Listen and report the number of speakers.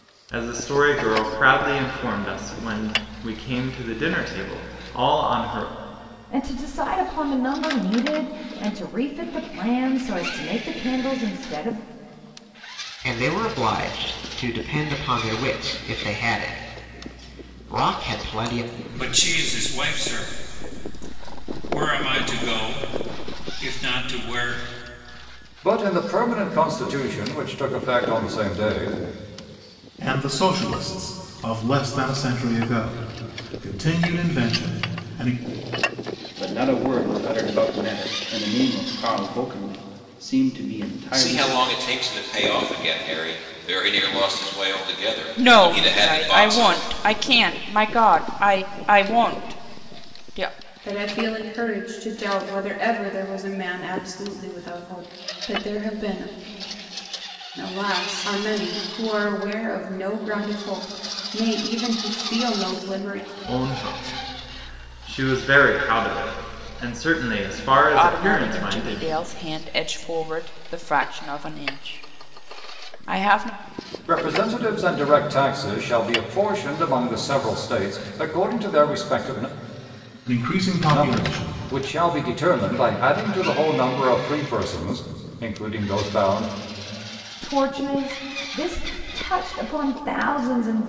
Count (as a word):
ten